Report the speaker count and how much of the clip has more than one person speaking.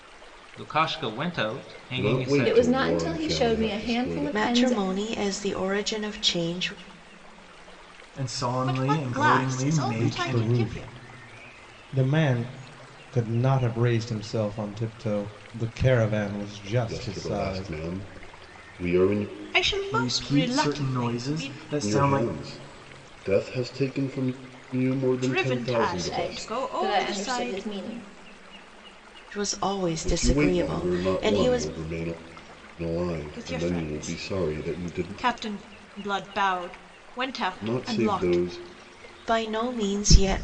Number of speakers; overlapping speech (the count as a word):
seven, about 38%